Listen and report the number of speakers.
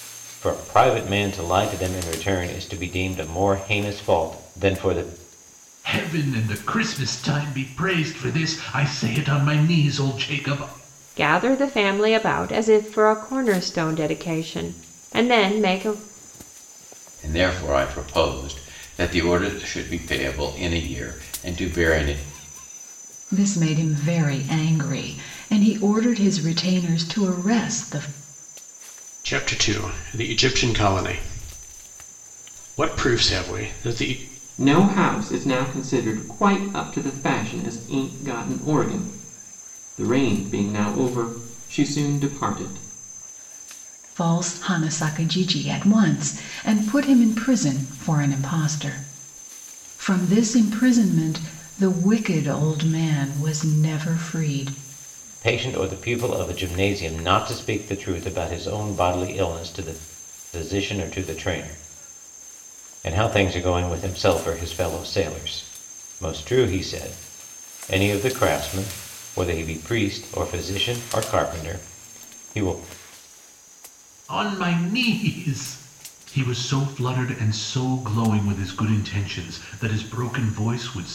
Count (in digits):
7